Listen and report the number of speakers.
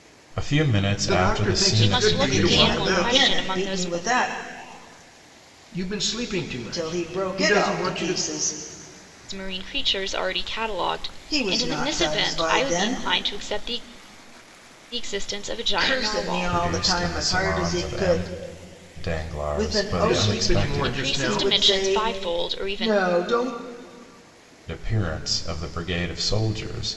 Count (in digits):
4